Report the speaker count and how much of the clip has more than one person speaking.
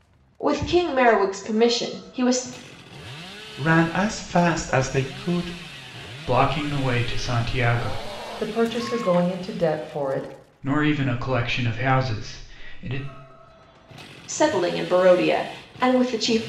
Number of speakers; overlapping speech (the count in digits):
4, no overlap